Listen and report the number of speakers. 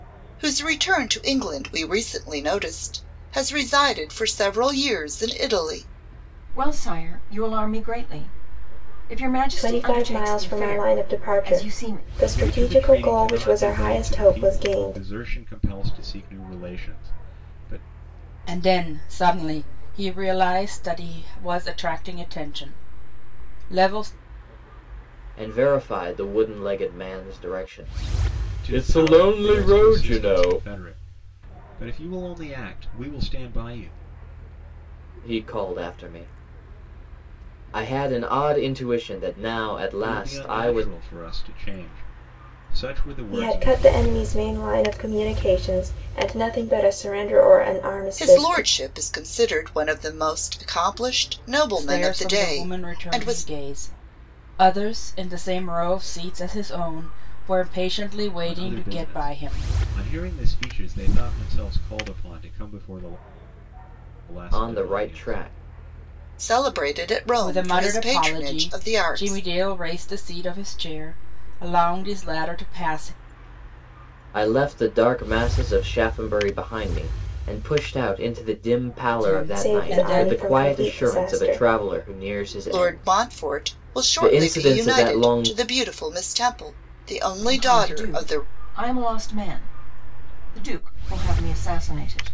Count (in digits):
6